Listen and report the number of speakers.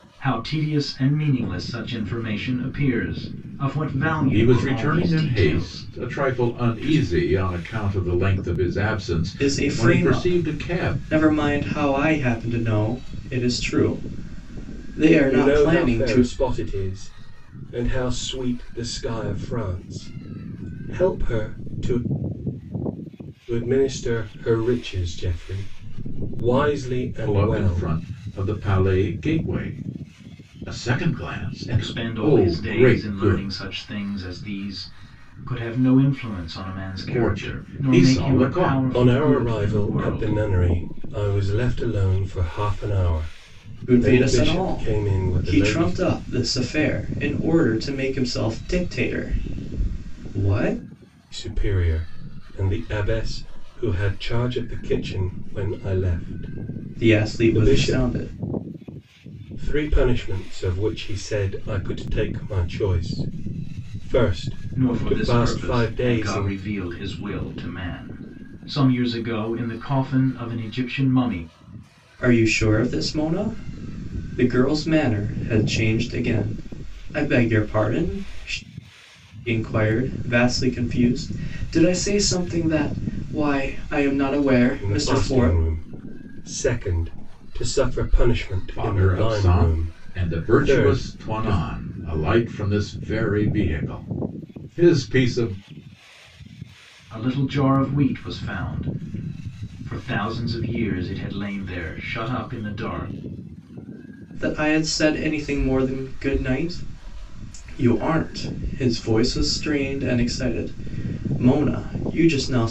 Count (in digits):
4